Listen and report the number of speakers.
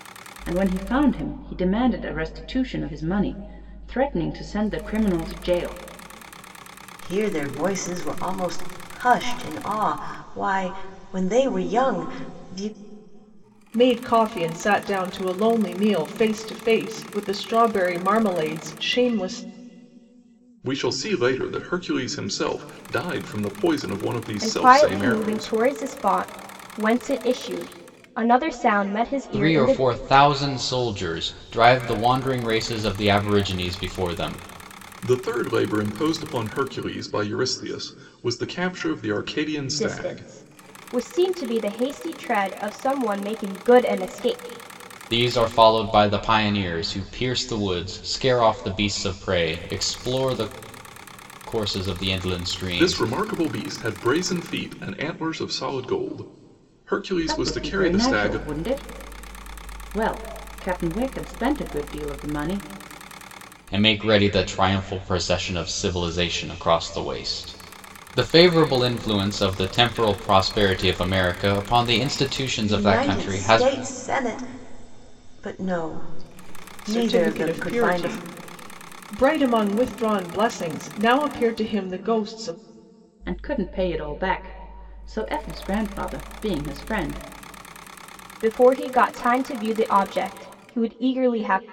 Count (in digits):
6